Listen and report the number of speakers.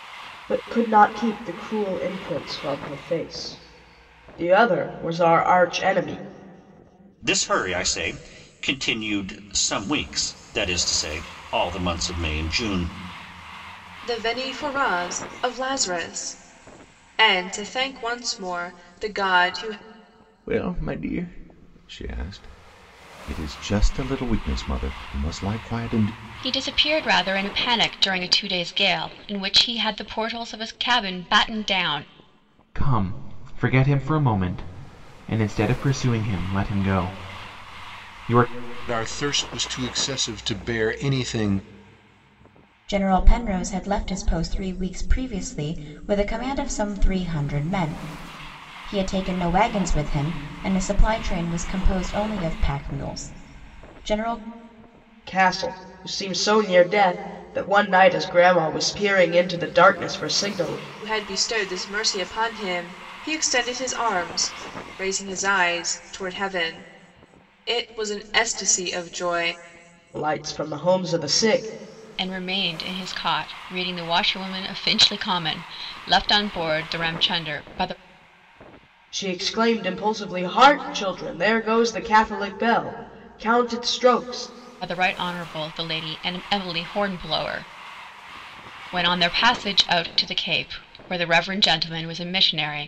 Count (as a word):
eight